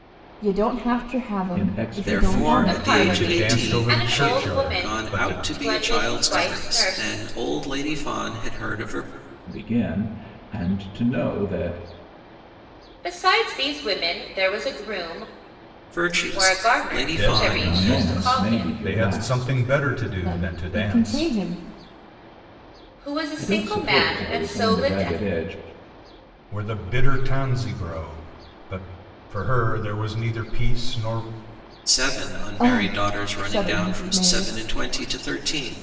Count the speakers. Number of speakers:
5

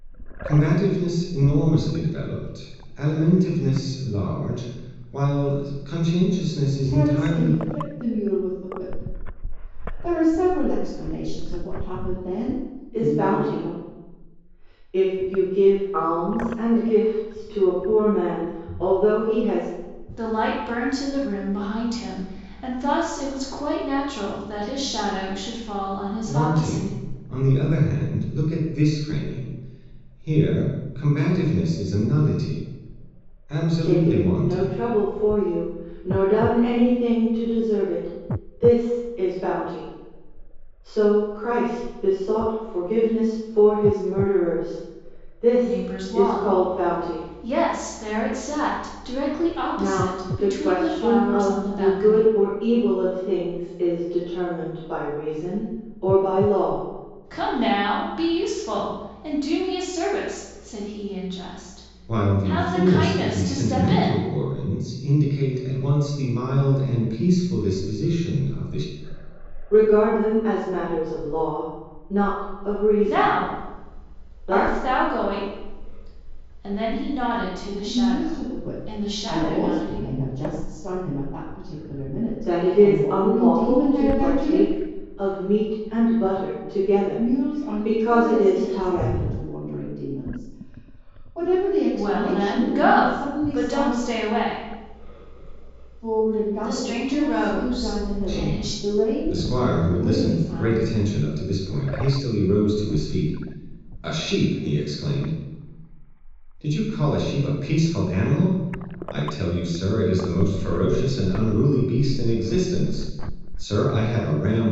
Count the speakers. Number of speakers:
4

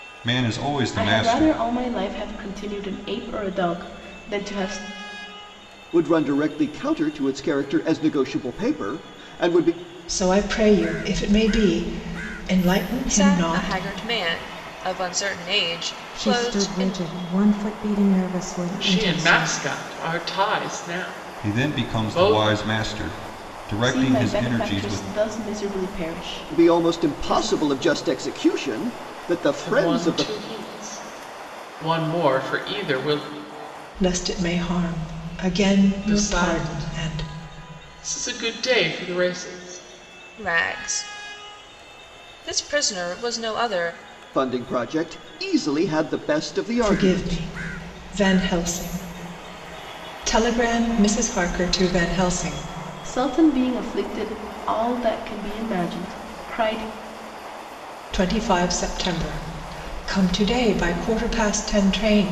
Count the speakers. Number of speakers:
7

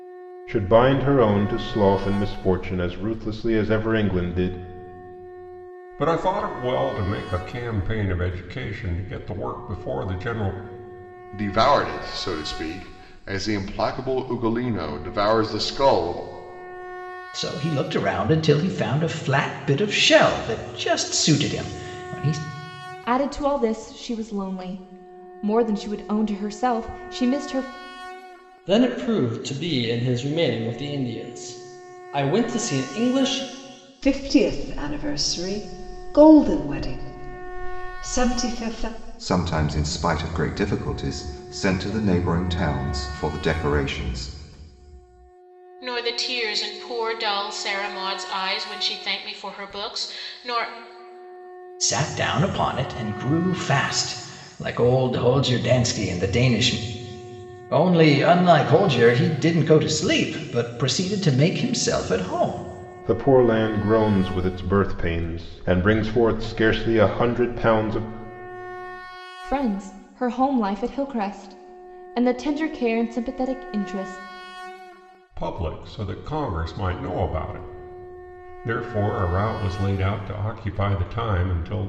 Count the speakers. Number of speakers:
9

